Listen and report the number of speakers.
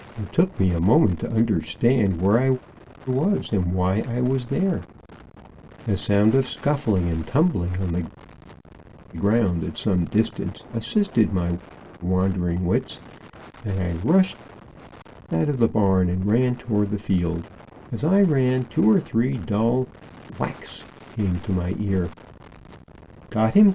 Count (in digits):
1